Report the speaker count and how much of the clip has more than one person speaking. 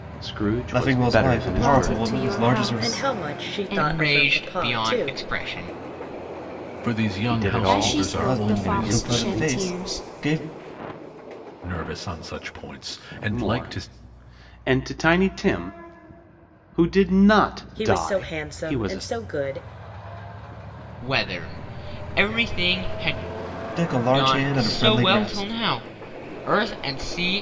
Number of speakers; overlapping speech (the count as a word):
six, about 39%